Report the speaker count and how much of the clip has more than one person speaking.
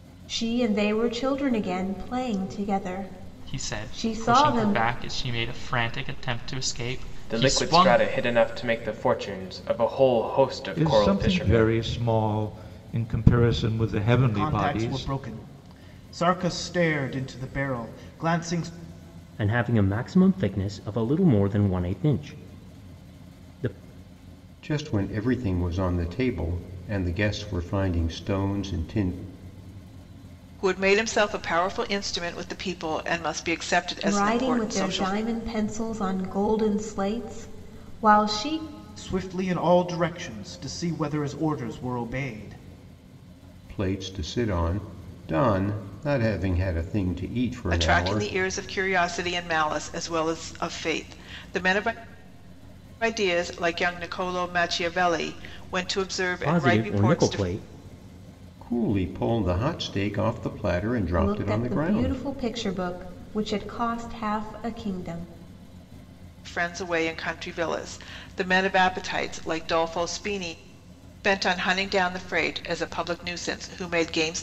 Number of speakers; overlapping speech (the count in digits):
8, about 11%